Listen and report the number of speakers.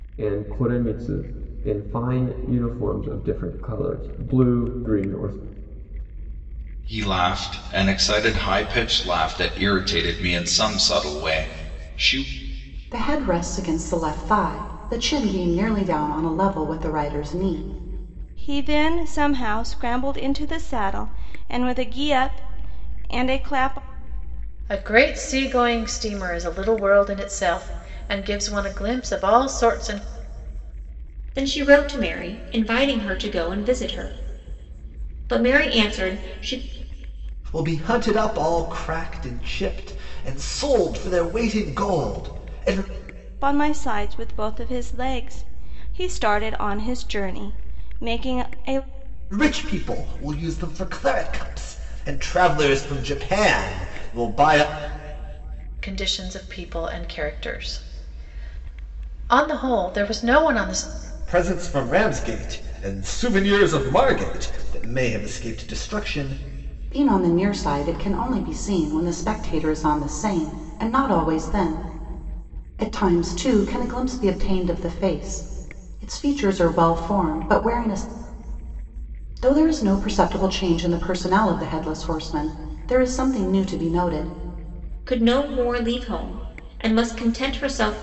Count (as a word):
seven